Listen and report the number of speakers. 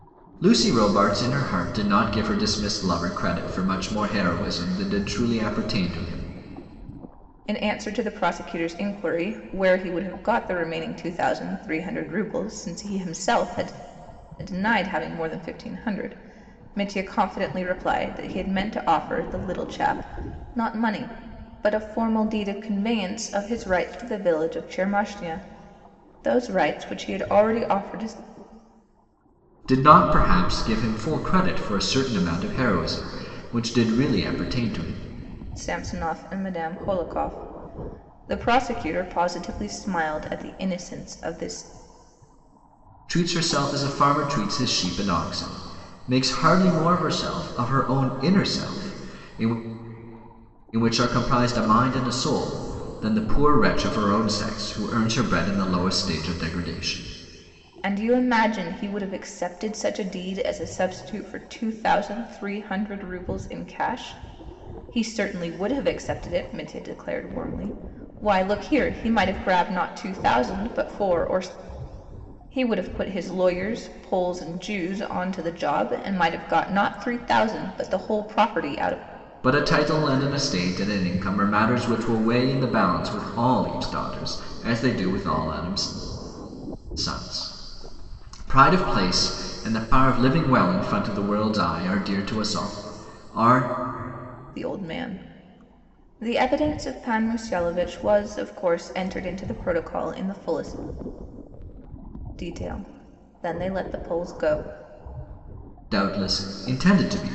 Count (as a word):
two